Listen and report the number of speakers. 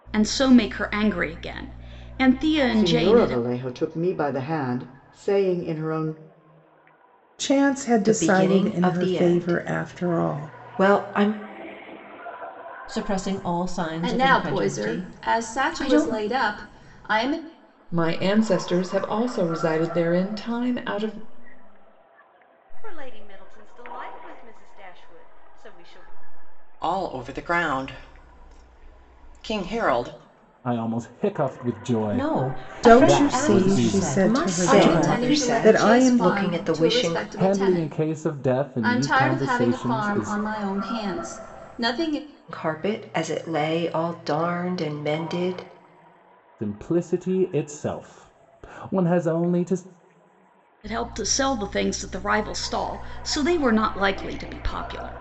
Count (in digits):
10